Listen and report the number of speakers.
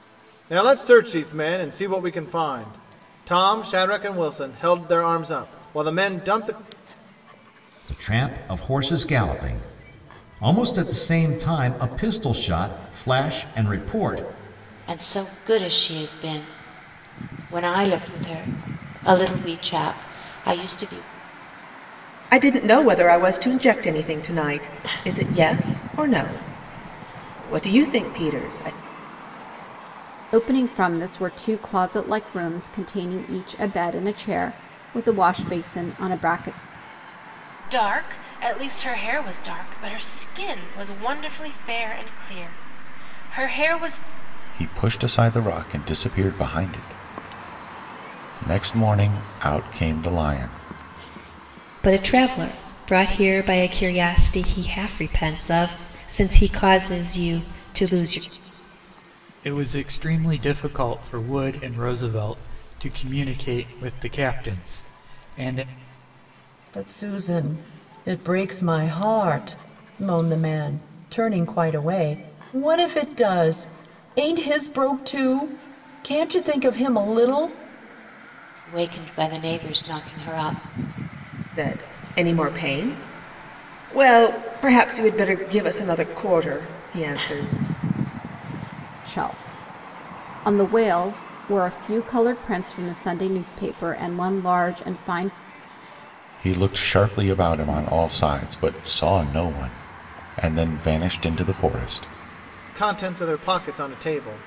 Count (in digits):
10